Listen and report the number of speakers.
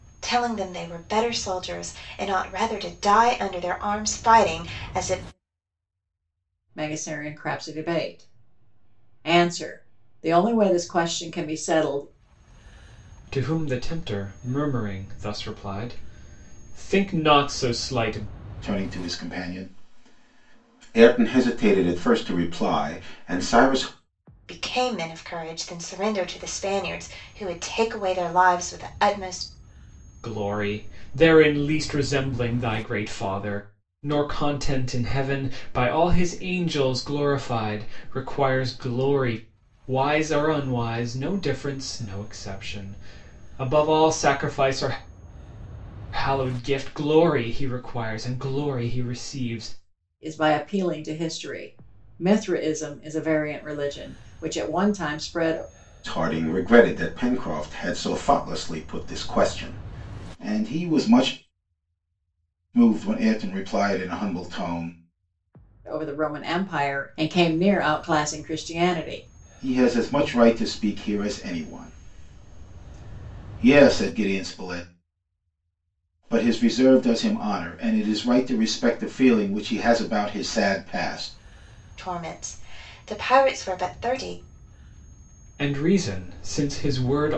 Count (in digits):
4